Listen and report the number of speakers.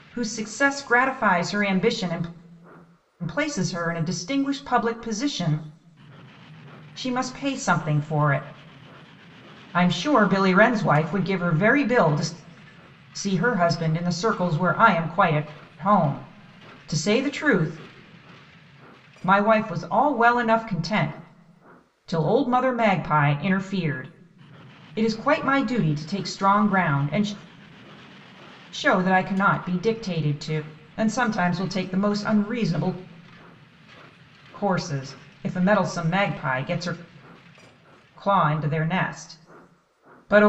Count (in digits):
1